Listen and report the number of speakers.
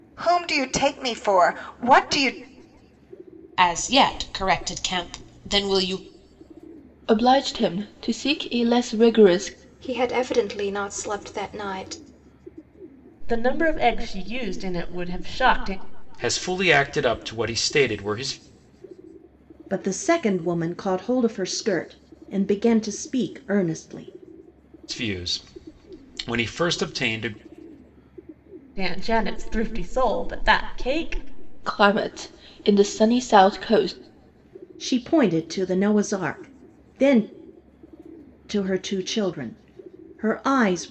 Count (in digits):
7